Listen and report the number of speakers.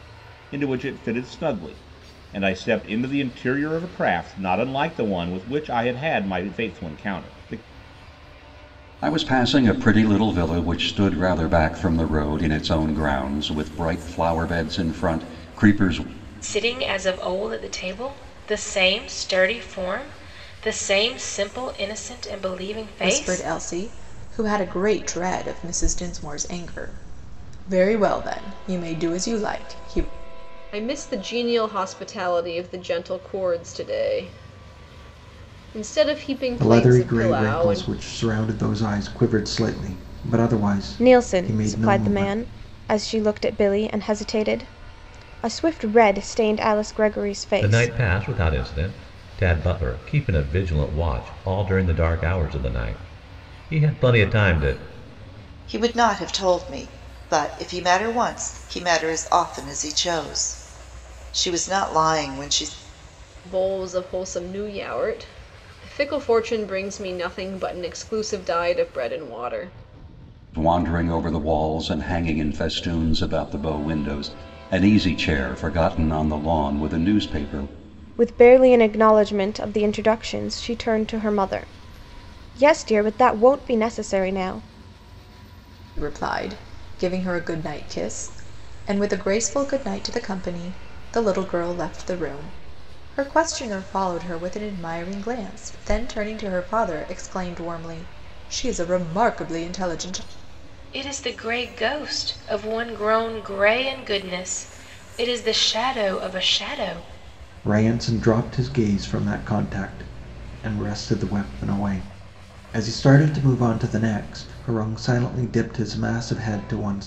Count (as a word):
nine